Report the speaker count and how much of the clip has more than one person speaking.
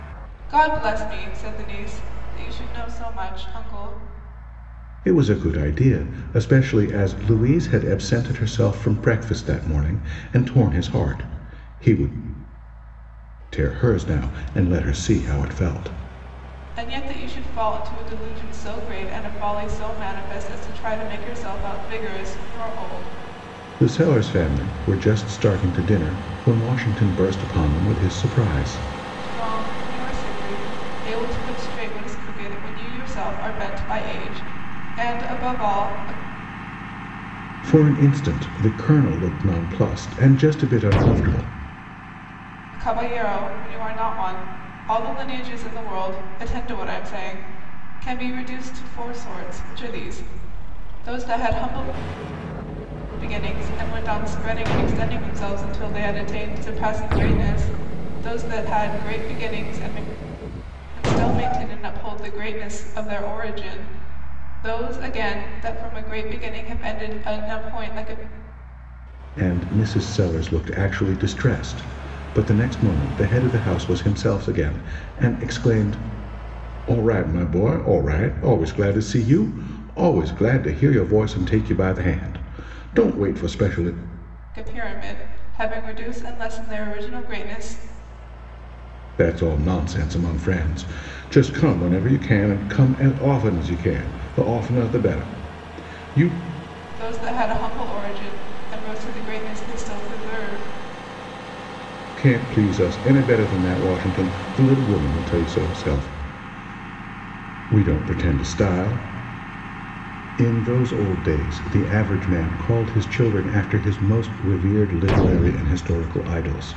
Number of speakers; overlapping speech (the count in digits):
2, no overlap